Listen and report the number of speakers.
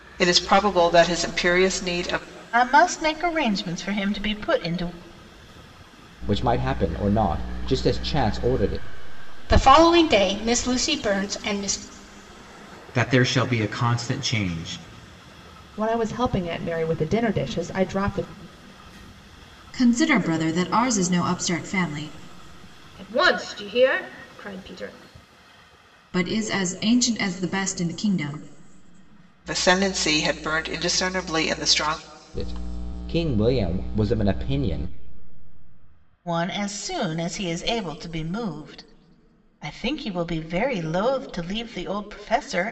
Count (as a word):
eight